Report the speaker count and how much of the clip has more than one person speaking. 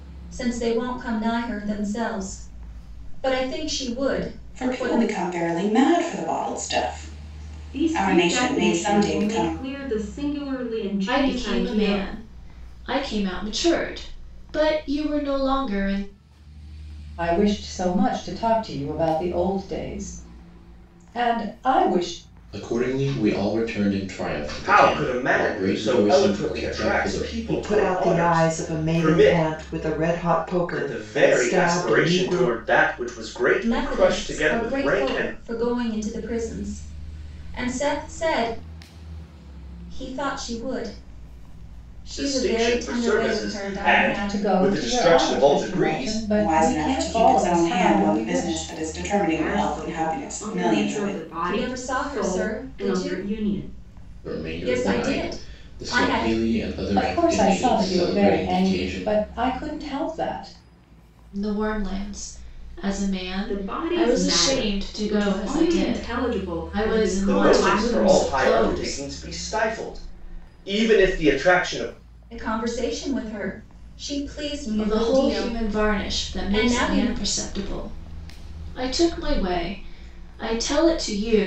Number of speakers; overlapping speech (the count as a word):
eight, about 42%